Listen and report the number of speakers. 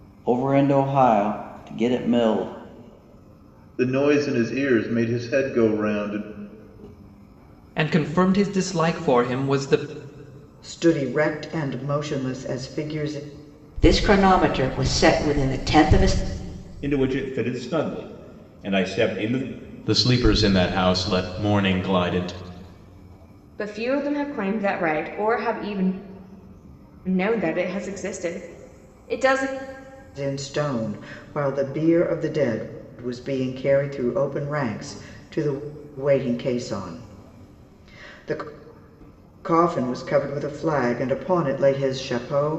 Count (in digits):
8